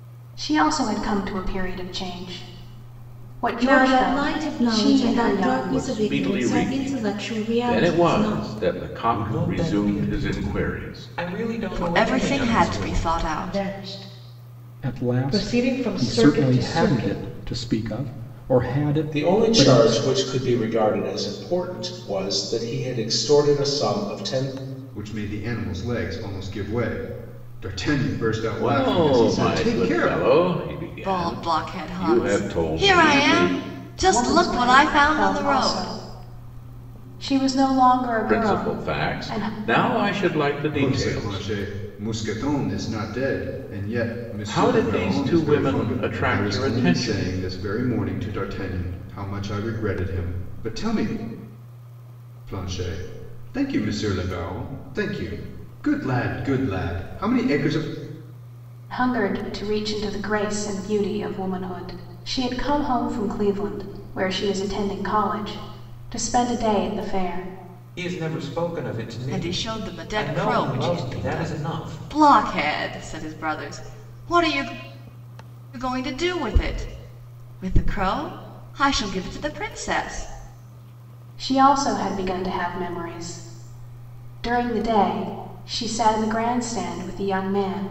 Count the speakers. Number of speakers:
9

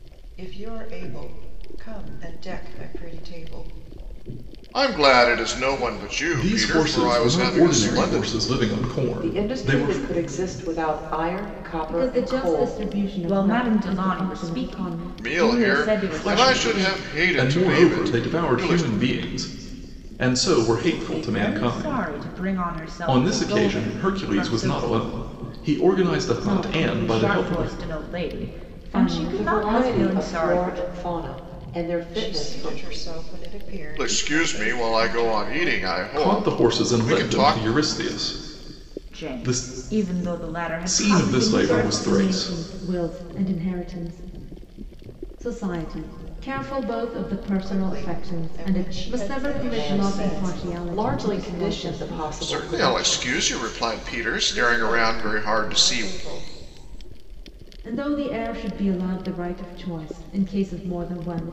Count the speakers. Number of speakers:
6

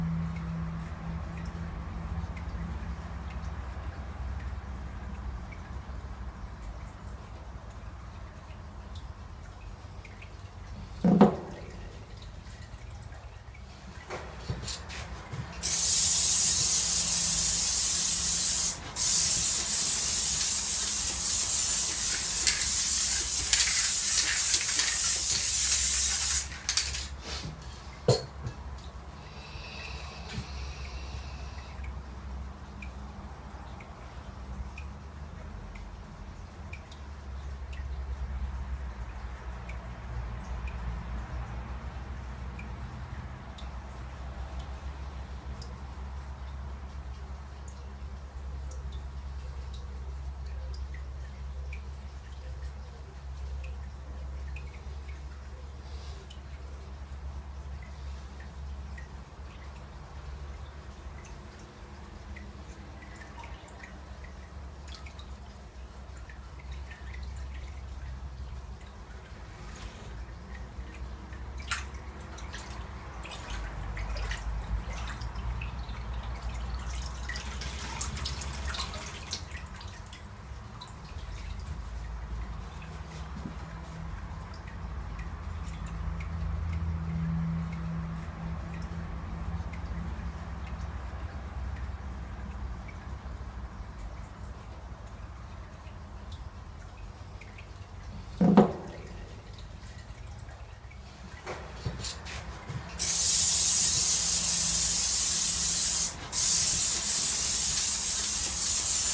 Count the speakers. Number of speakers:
0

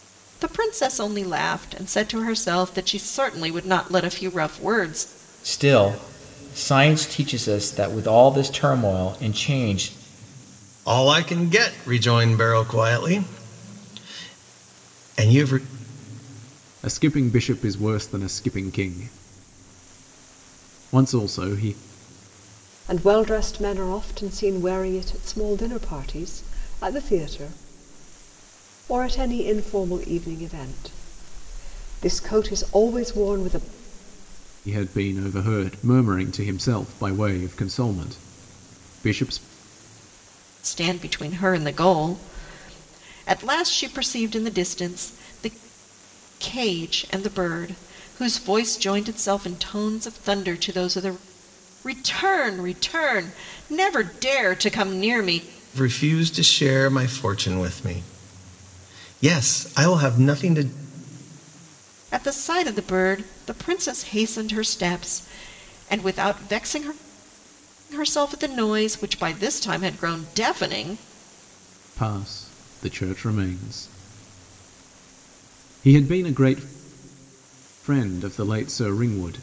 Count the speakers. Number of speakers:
5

